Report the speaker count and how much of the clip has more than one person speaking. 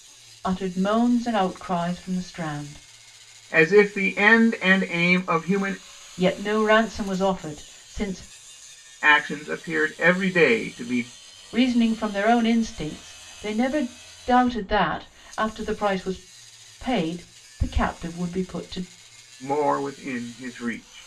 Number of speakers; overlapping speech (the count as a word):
two, no overlap